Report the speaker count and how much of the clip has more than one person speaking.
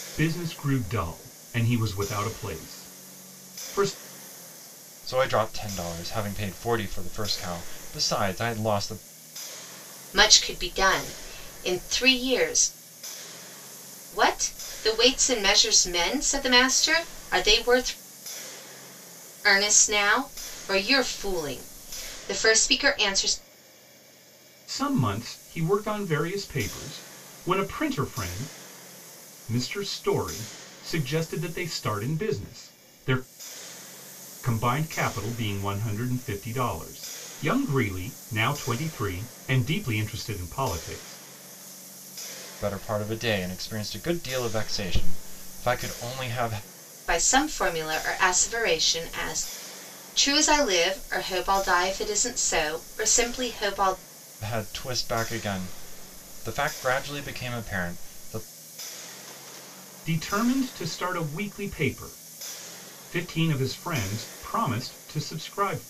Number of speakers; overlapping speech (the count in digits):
3, no overlap